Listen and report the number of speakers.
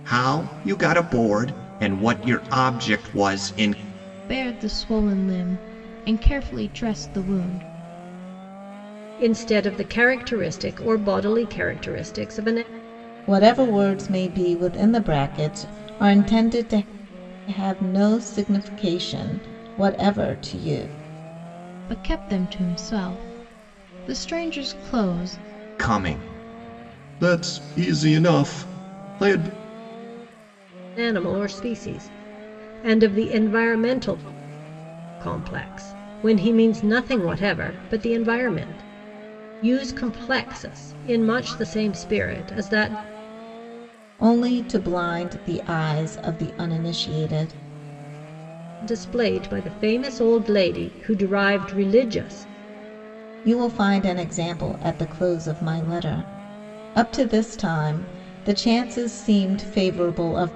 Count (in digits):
4